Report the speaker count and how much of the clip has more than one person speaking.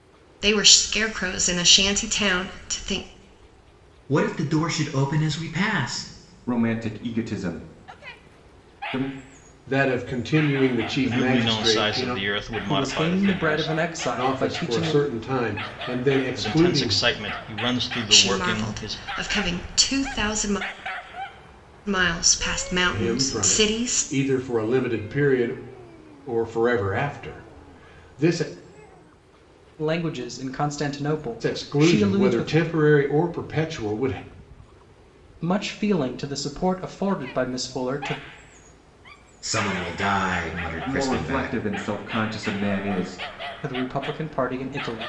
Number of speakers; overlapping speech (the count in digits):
6, about 17%